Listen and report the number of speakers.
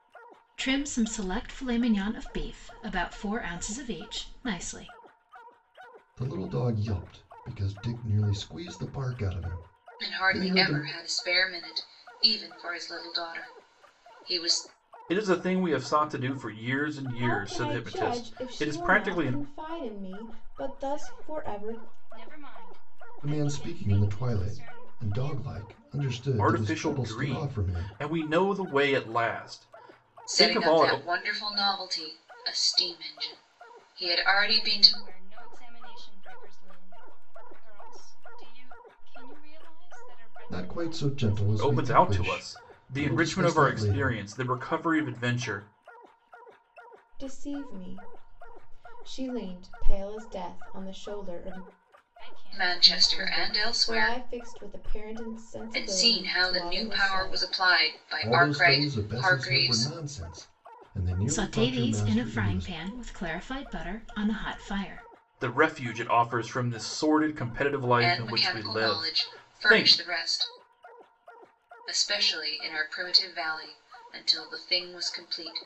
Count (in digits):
6